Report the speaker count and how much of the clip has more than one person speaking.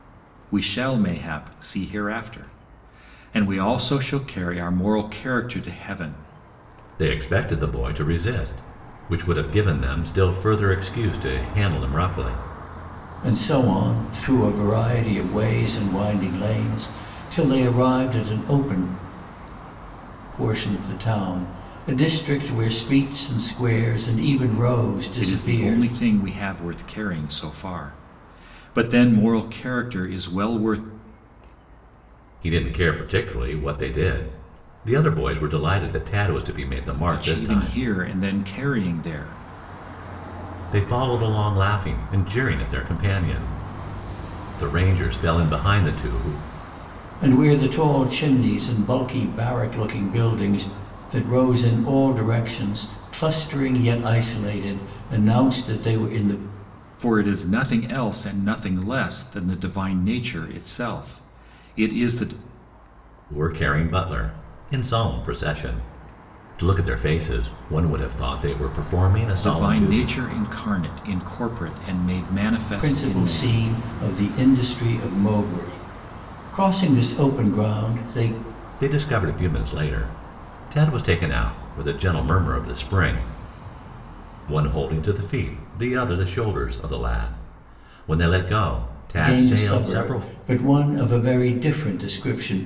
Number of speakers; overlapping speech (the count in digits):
3, about 5%